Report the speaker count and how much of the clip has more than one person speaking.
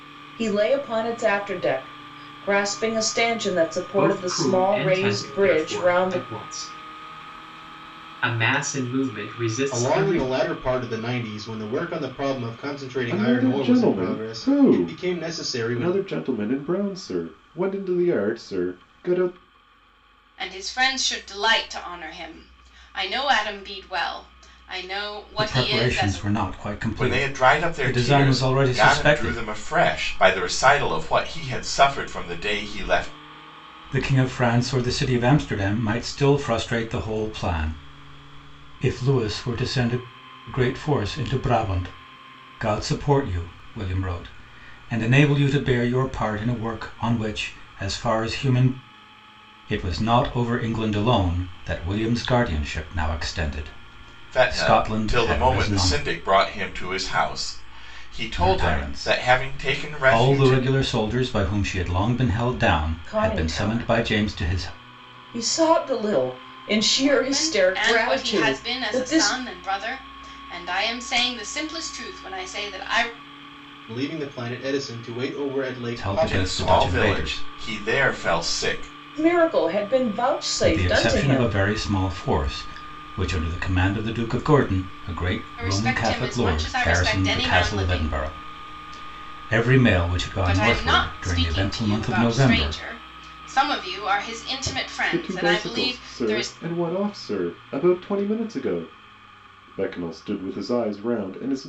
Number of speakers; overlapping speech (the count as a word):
seven, about 26%